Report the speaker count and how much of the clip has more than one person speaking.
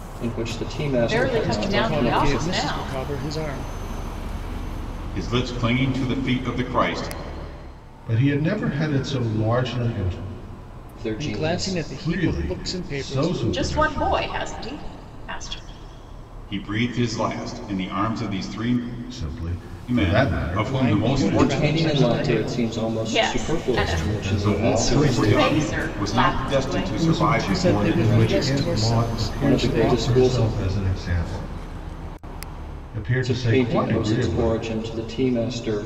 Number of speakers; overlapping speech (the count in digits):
5, about 46%